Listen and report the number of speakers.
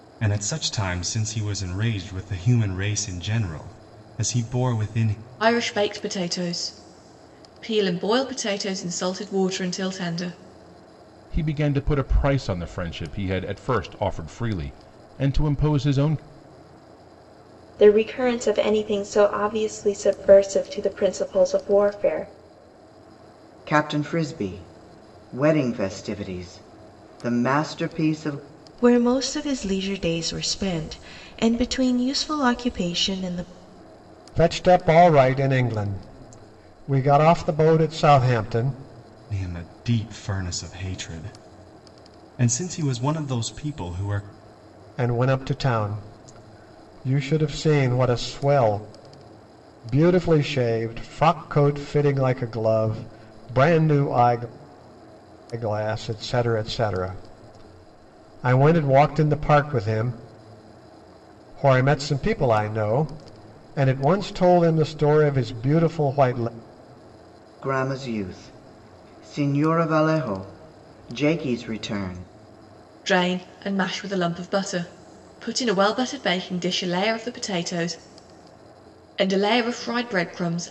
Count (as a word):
seven